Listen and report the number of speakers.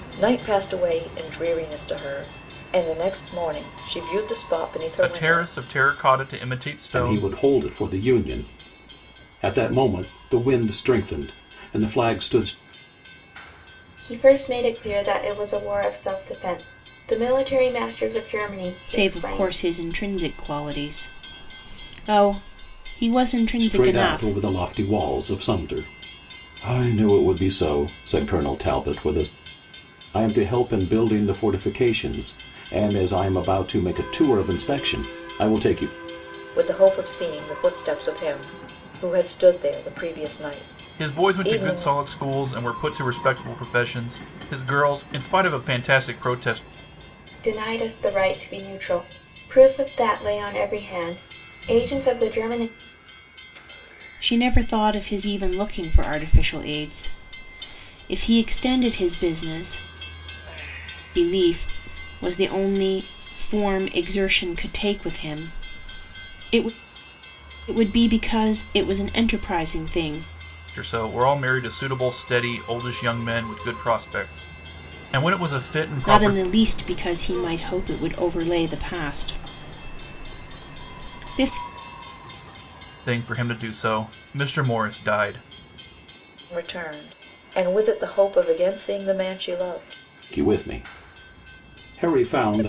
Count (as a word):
five